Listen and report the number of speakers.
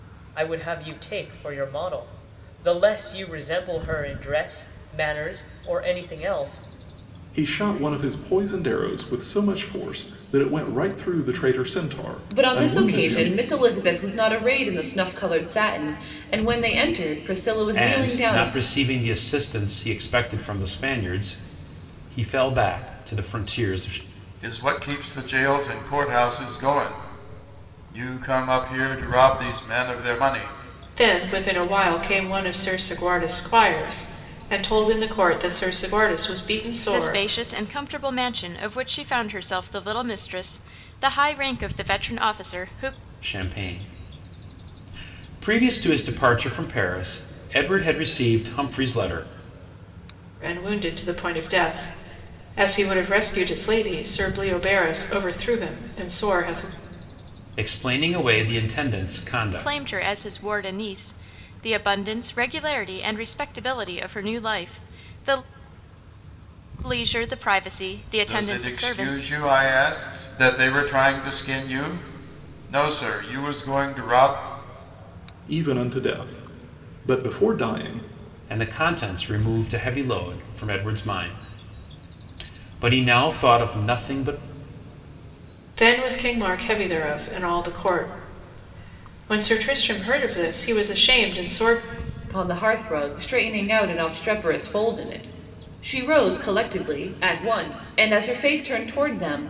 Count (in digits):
7